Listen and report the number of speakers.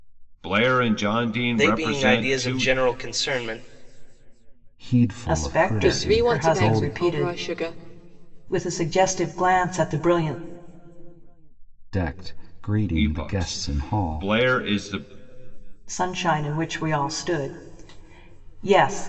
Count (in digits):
5